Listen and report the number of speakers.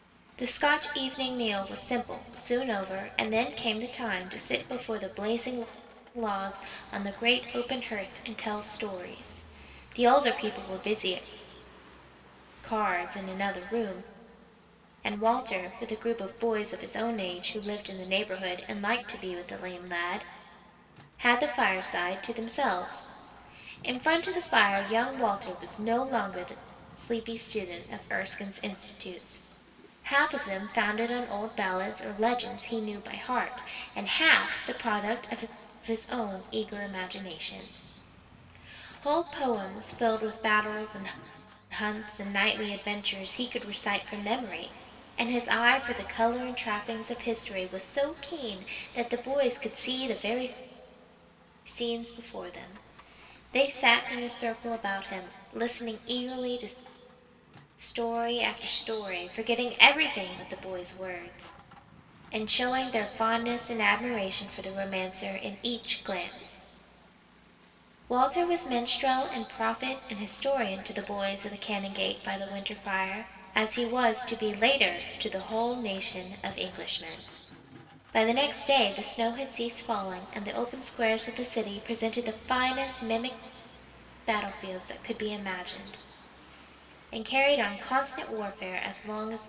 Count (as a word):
one